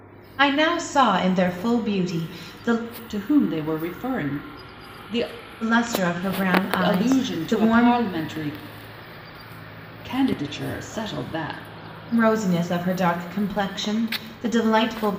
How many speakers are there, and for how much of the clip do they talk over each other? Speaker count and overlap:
2, about 8%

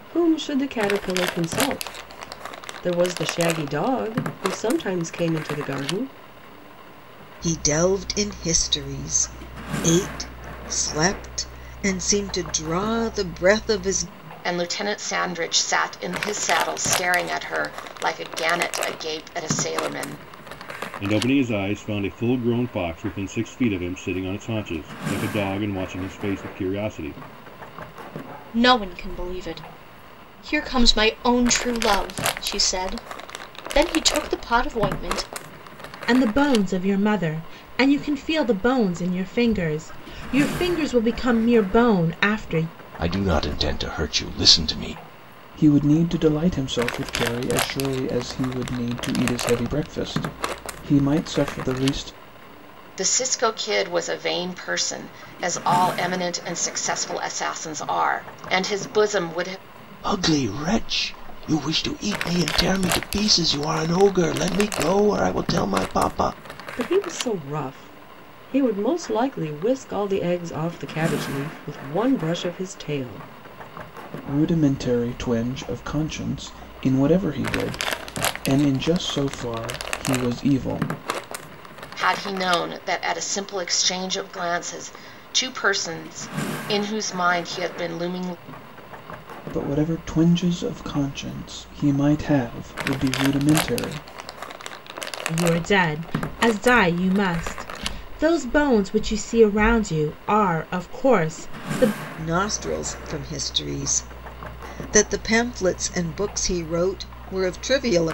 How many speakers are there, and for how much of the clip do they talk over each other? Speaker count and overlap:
8, no overlap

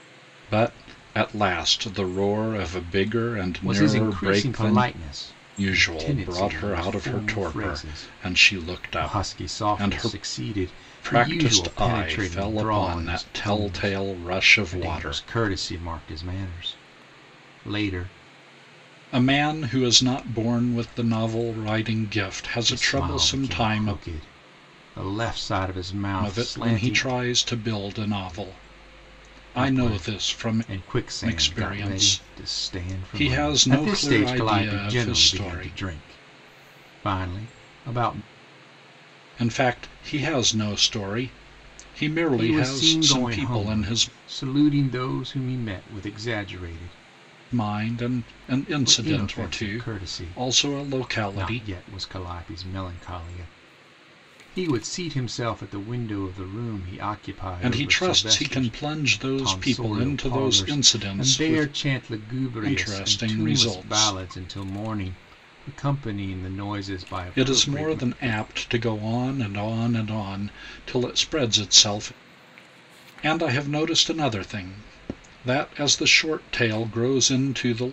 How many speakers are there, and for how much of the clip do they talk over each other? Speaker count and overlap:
2, about 36%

